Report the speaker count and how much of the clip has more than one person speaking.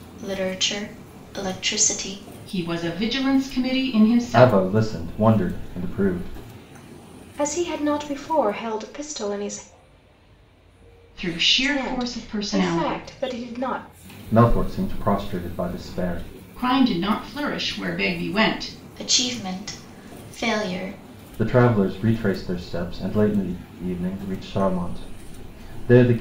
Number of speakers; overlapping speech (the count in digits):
4, about 7%